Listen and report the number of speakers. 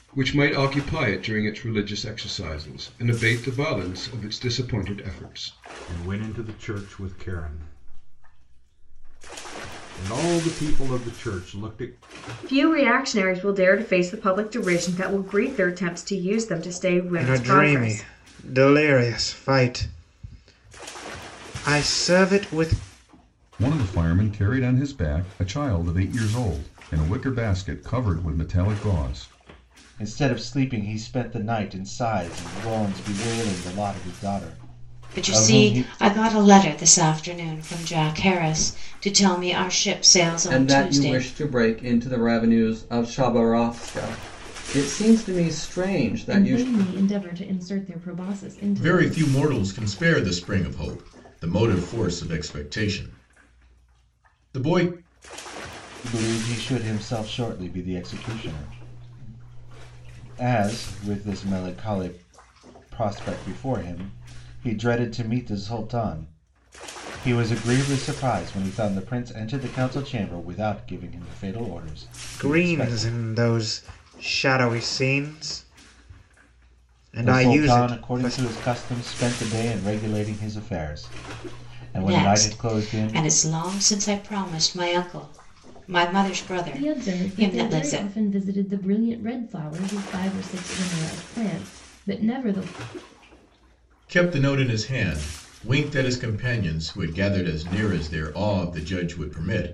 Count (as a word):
ten